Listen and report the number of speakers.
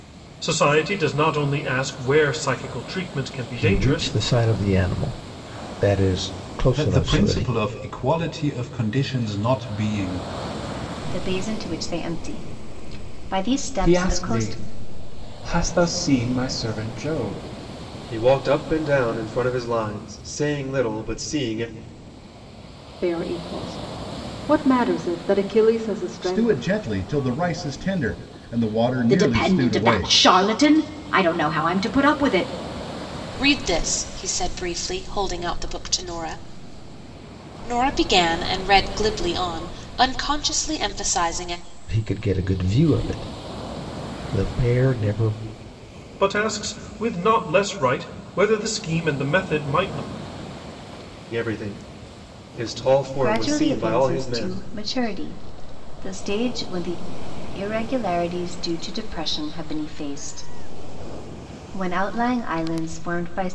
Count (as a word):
ten